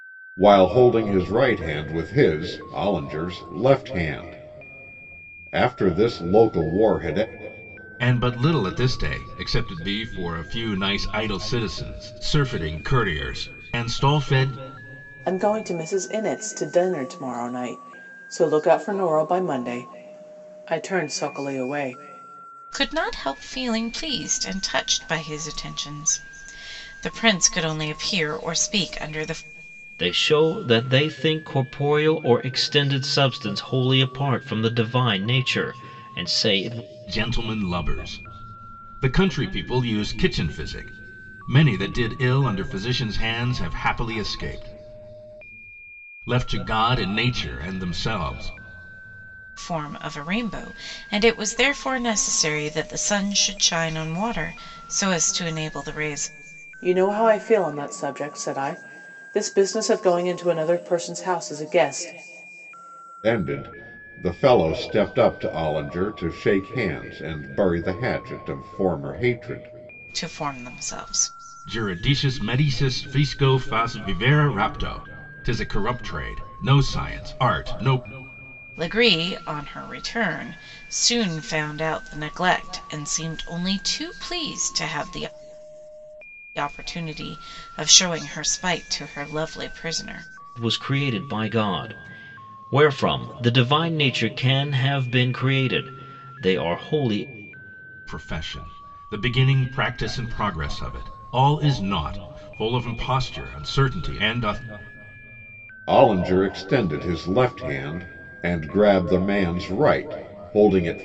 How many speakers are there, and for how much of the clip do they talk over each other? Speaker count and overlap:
5, no overlap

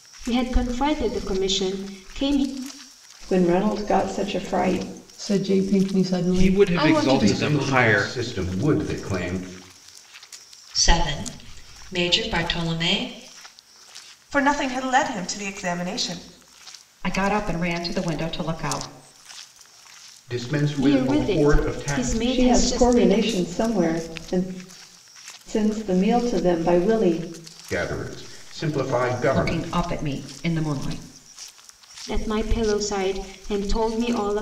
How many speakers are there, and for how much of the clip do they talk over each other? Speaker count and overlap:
8, about 13%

